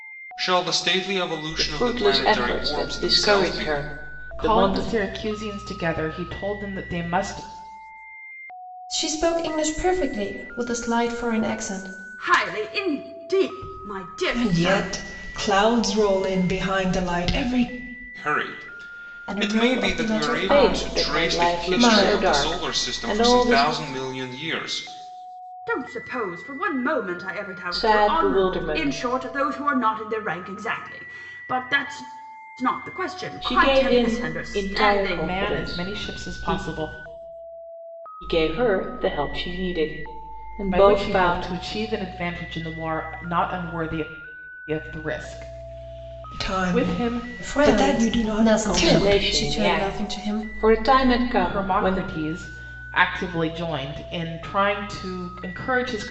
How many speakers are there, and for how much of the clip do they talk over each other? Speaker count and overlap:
6, about 32%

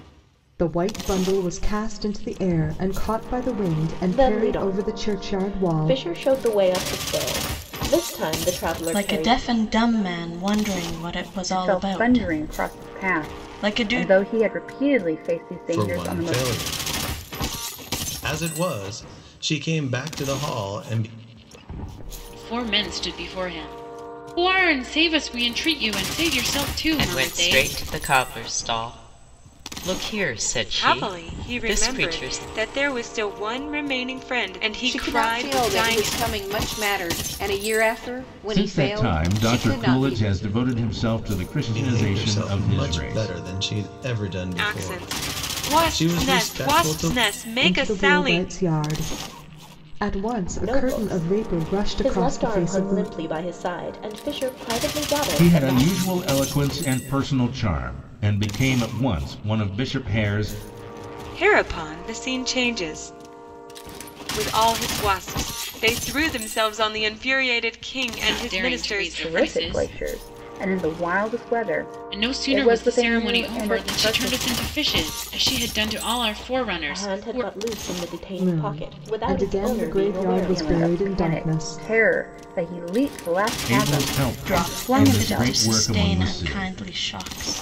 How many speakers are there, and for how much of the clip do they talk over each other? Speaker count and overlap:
10, about 35%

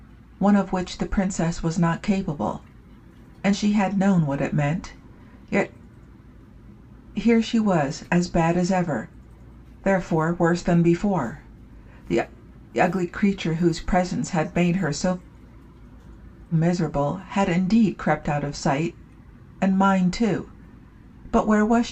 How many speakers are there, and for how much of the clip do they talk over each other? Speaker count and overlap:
1, no overlap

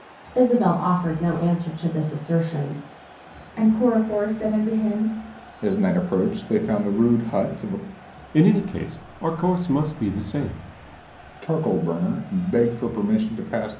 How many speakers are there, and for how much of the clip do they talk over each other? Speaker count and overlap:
4, no overlap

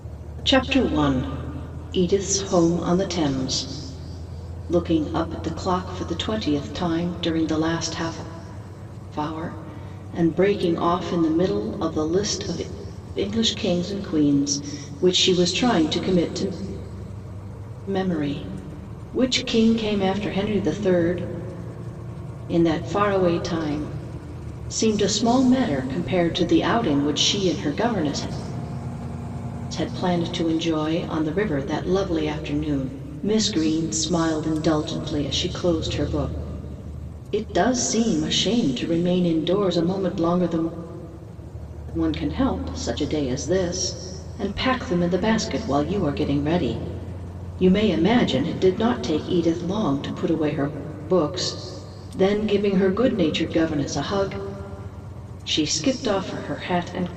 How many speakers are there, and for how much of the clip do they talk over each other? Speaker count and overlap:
1, no overlap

